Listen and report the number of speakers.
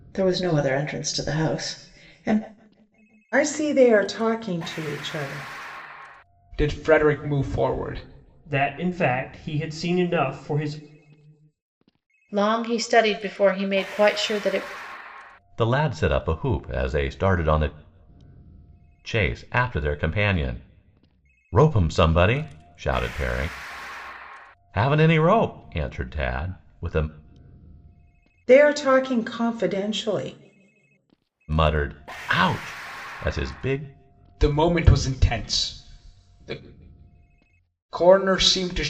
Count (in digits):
6